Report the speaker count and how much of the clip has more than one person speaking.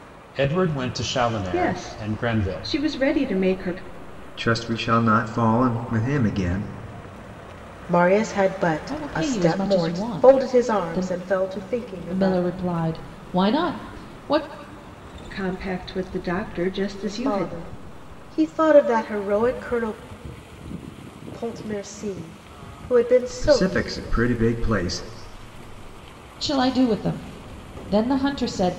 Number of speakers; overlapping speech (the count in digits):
5, about 17%